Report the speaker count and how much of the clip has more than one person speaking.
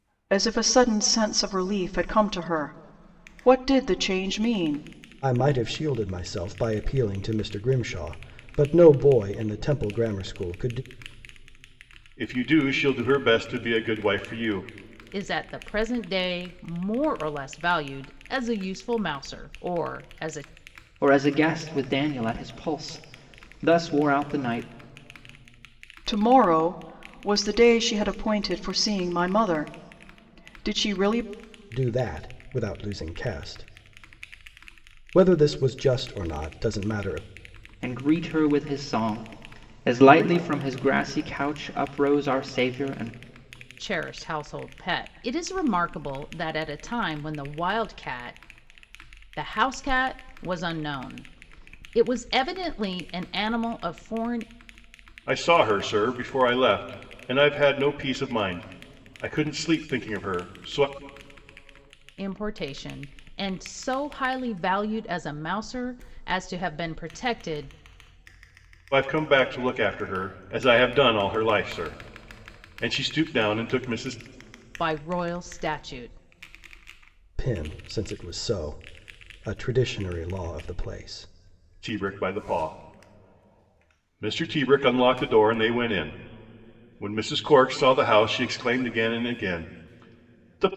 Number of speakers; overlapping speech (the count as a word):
five, no overlap